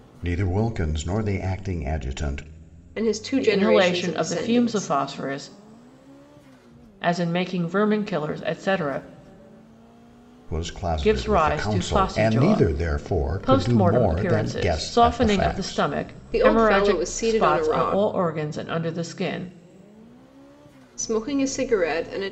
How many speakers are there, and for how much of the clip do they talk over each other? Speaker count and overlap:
three, about 34%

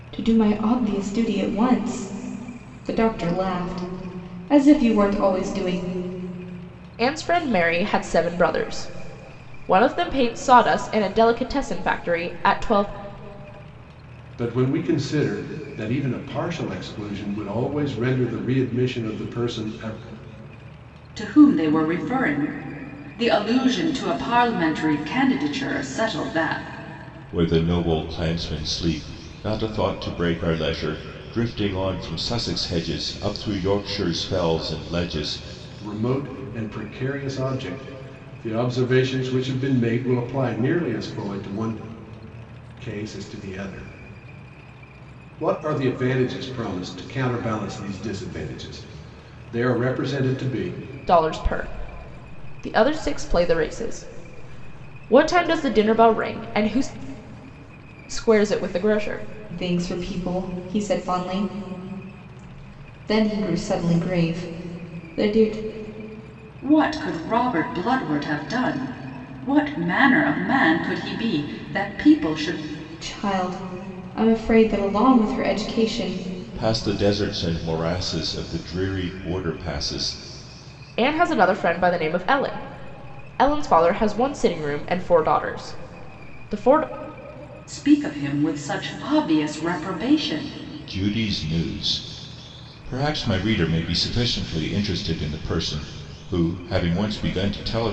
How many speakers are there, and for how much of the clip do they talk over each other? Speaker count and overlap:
five, no overlap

